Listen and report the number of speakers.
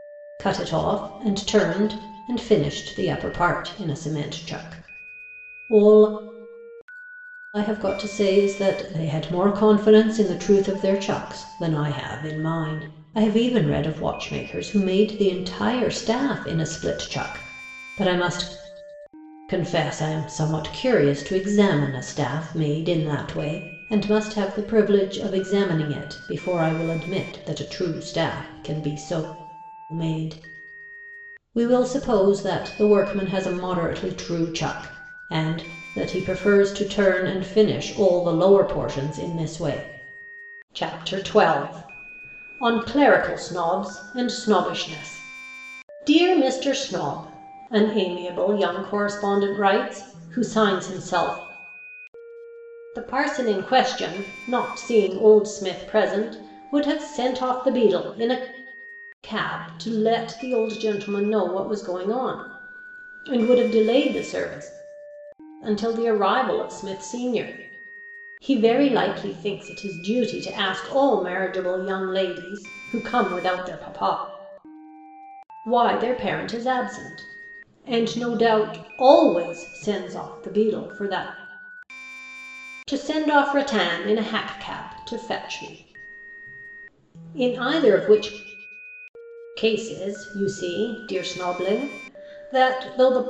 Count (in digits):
1